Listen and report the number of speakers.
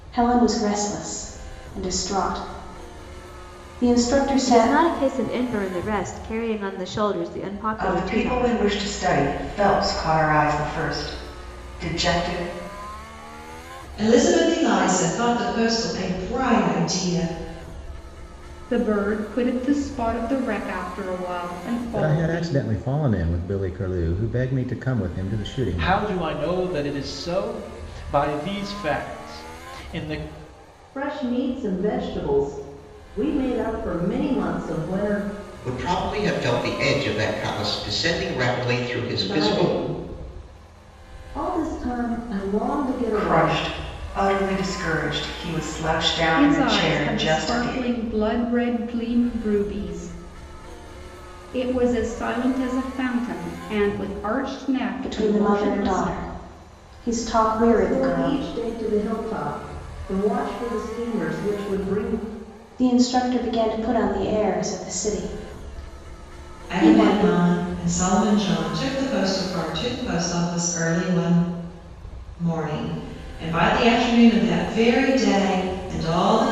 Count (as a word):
nine